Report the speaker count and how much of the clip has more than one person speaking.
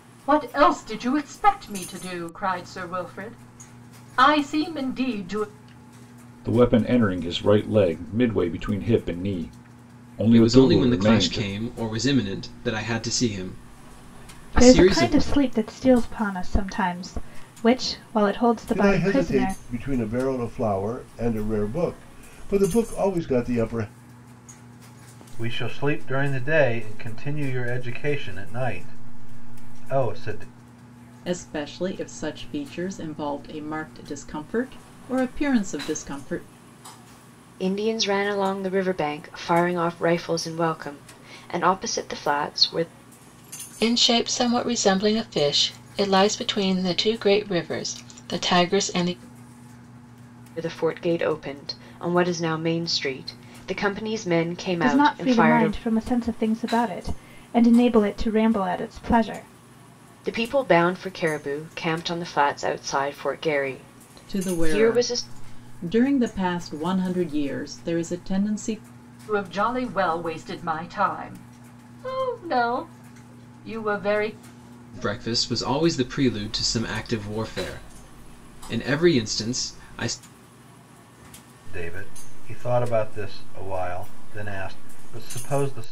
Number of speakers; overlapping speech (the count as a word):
nine, about 6%